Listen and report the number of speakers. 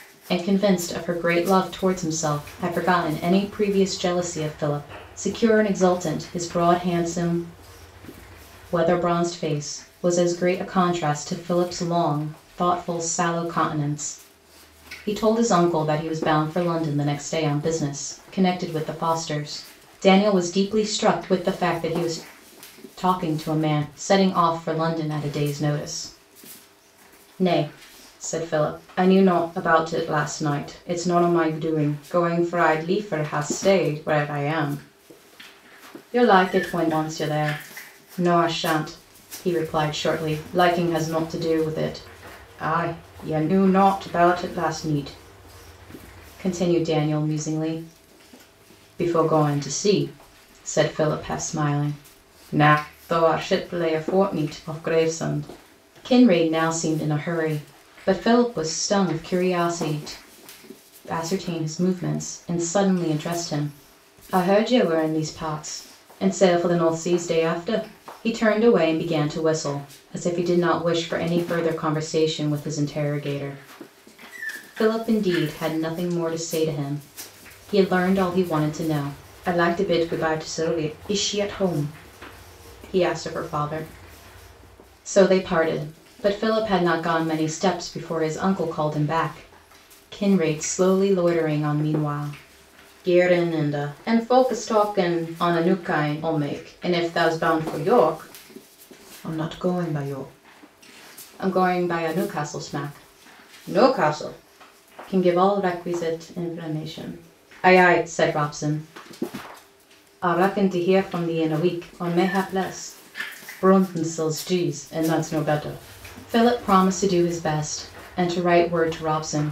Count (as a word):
one